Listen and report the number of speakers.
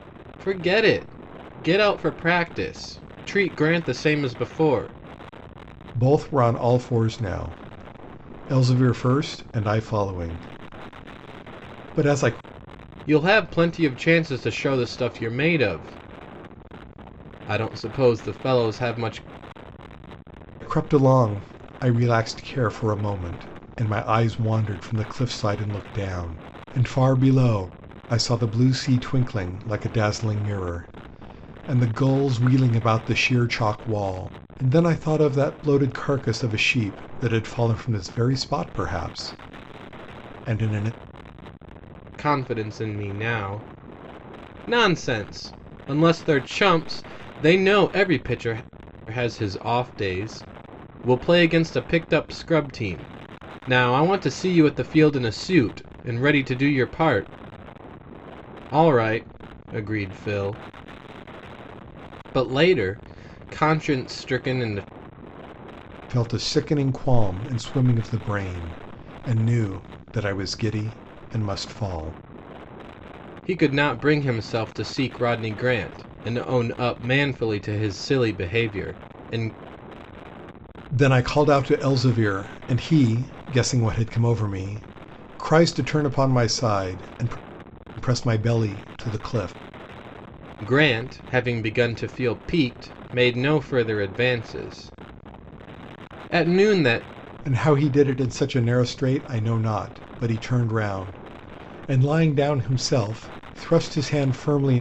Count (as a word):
two